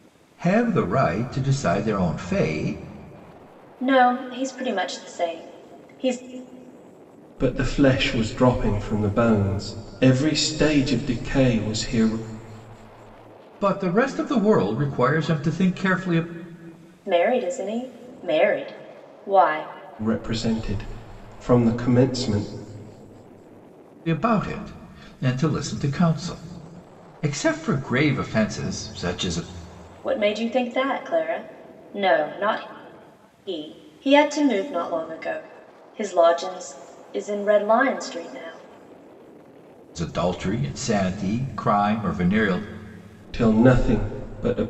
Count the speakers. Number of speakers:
three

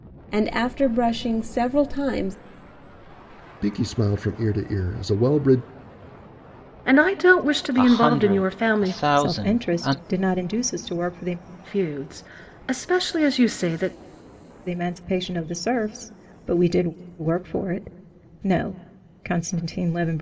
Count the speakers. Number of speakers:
five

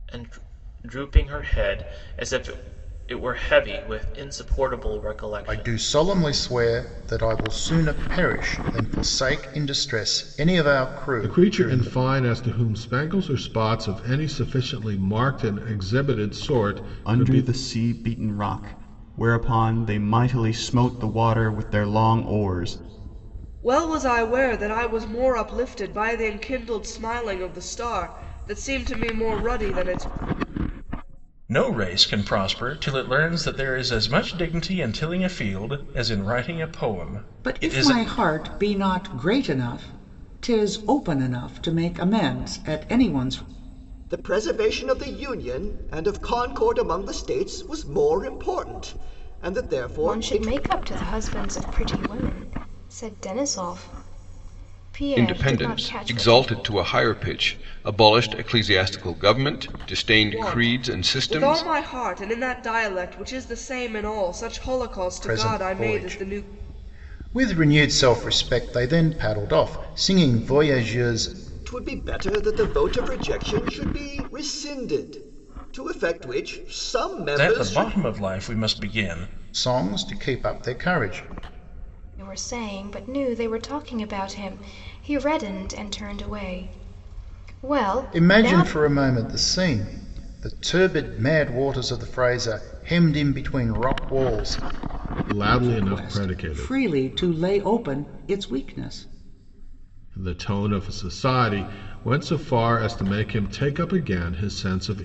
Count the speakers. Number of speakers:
ten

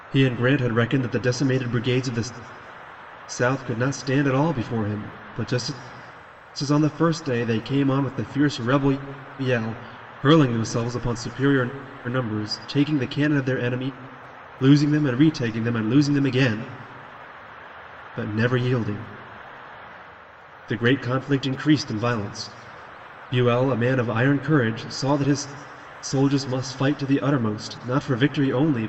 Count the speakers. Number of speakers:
one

